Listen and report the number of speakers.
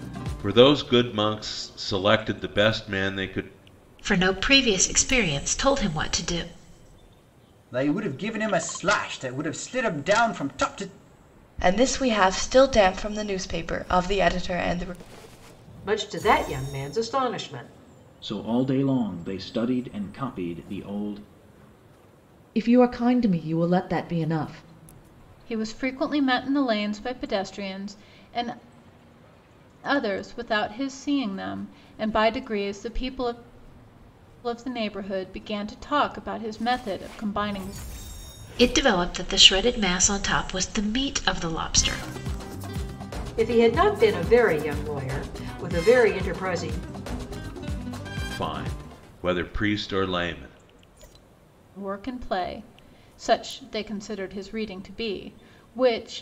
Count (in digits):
8